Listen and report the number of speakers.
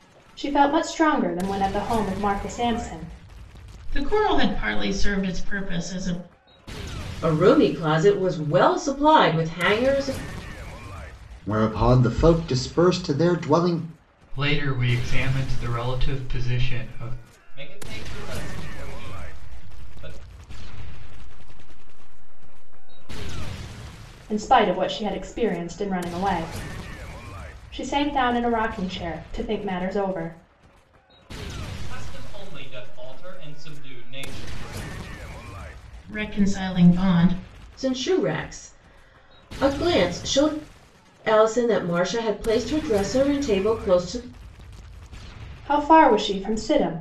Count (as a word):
seven